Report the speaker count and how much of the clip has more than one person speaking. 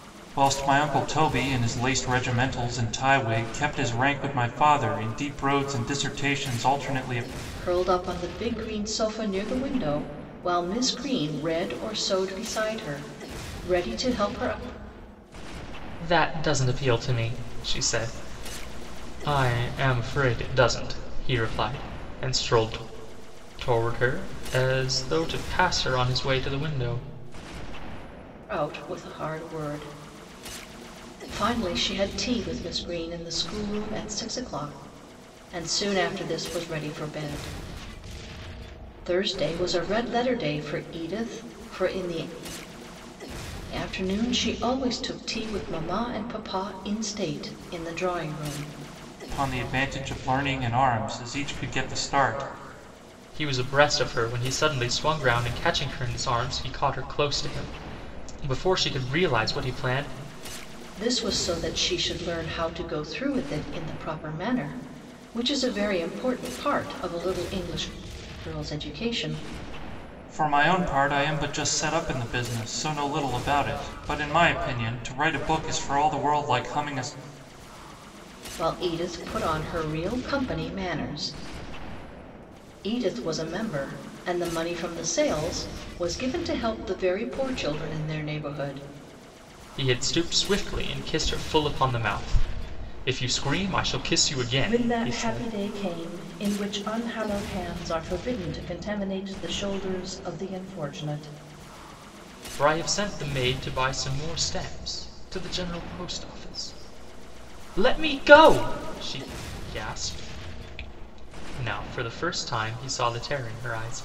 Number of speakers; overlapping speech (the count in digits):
3, about 1%